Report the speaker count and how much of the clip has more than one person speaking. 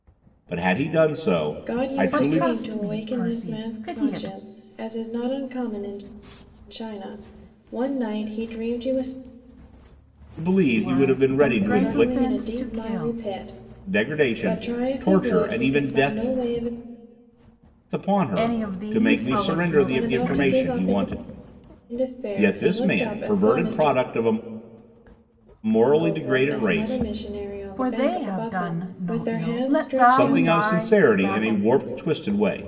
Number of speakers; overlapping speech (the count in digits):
3, about 51%